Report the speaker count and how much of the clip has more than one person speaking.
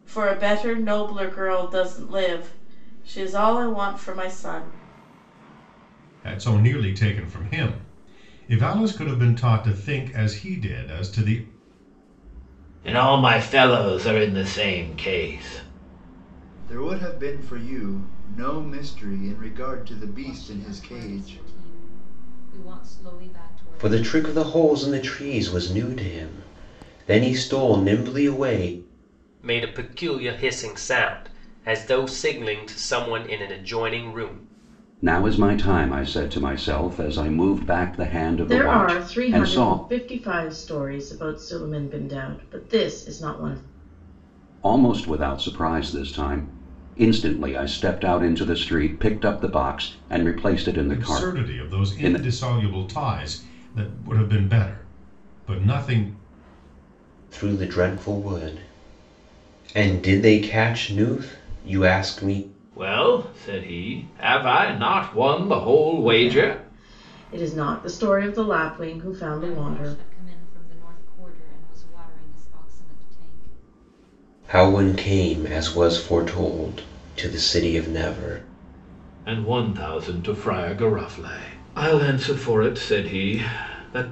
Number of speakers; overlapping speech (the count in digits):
8, about 7%